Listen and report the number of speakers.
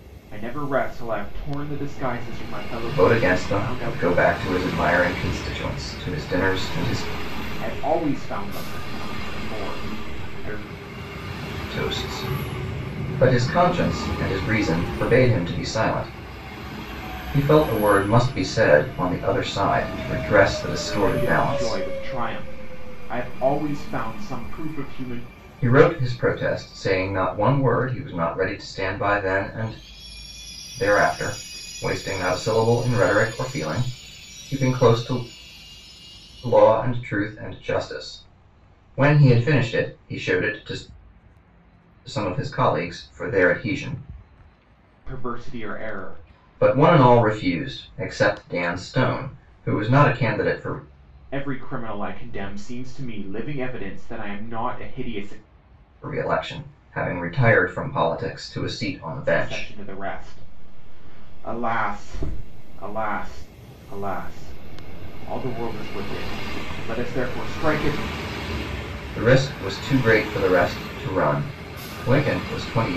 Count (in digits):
2